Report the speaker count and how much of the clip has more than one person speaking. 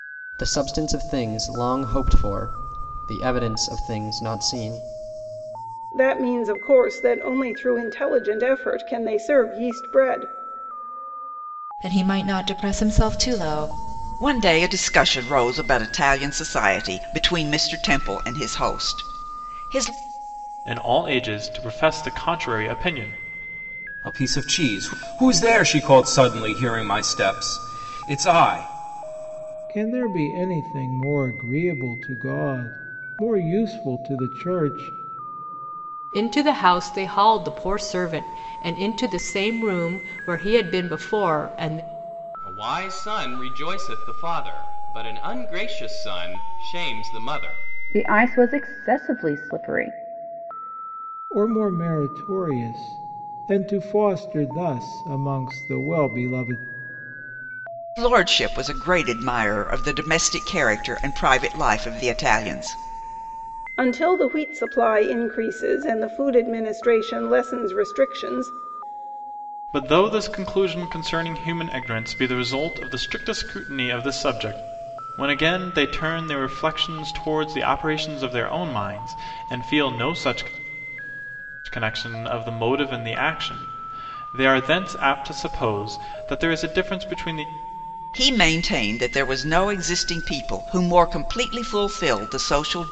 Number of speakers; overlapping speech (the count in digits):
10, no overlap